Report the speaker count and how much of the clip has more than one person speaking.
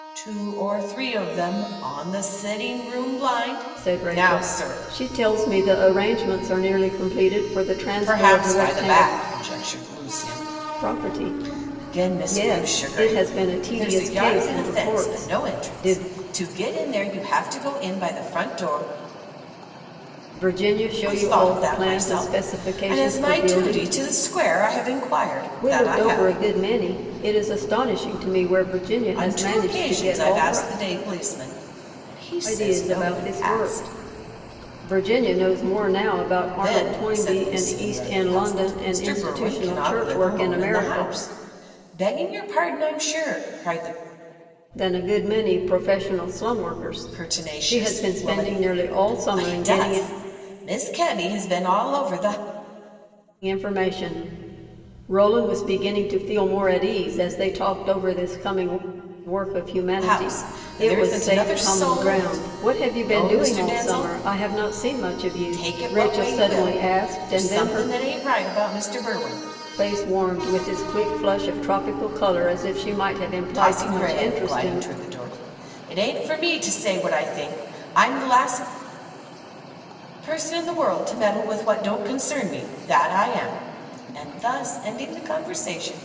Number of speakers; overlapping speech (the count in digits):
2, about 34%